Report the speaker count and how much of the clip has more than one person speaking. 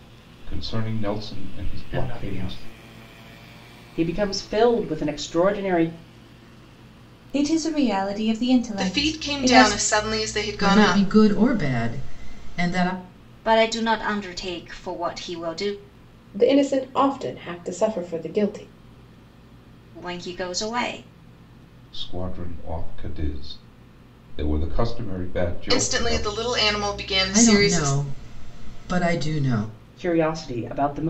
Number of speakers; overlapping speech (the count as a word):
eight, about 12%